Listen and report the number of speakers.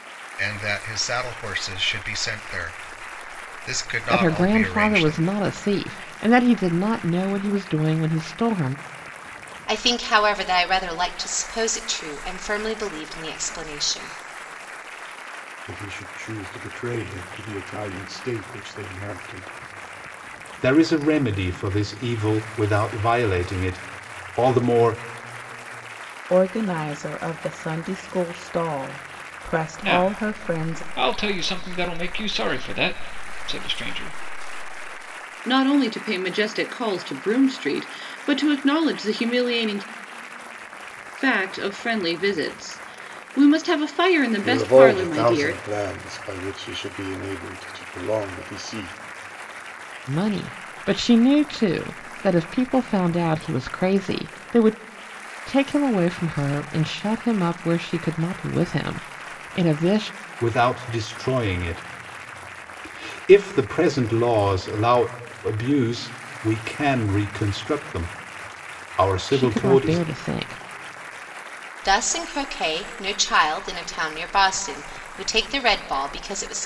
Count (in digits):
8